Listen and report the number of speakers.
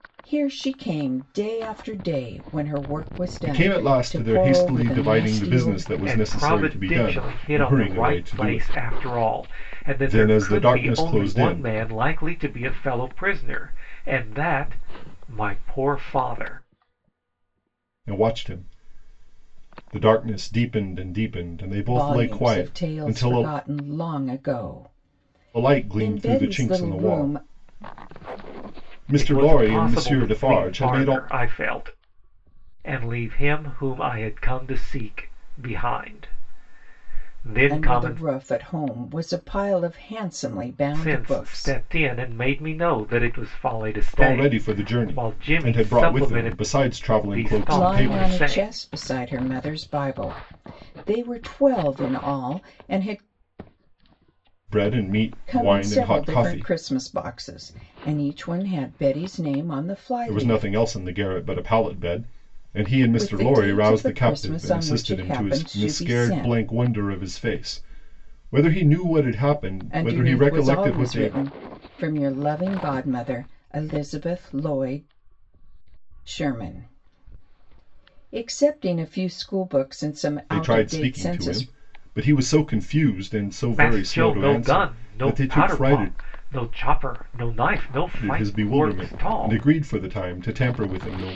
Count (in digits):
3